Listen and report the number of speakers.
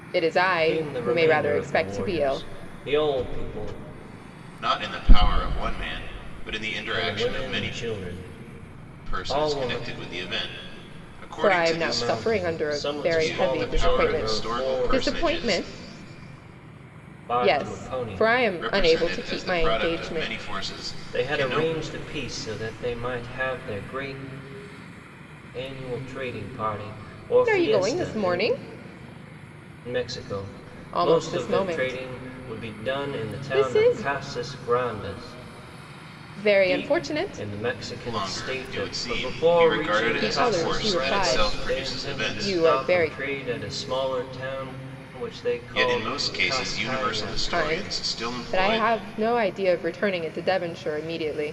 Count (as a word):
three